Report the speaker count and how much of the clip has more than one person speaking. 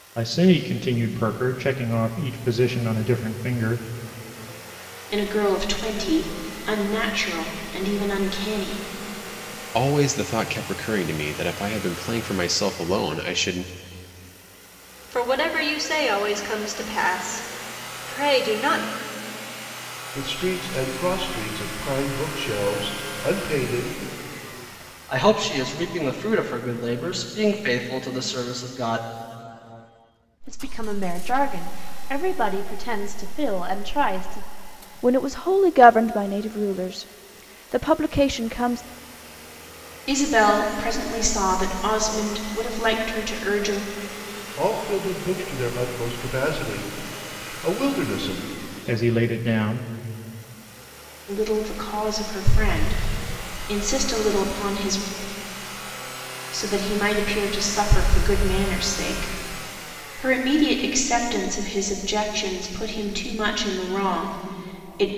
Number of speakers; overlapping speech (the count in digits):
8, no overlap